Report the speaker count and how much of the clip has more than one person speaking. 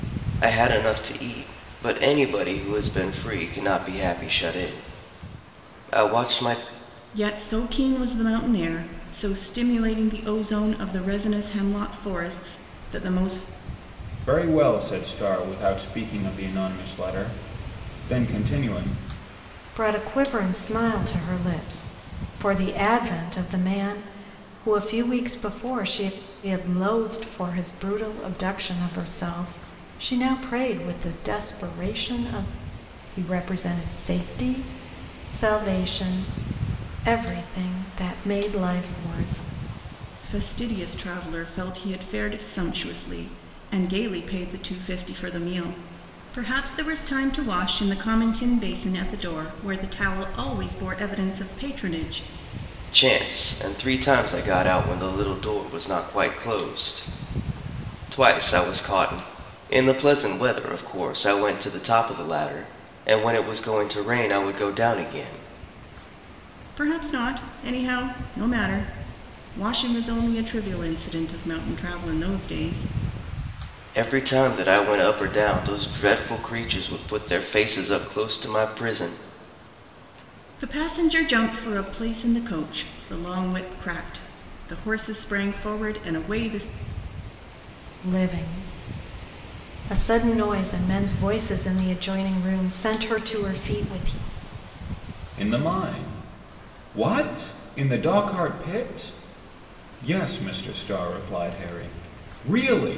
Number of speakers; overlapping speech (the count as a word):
four, no overlap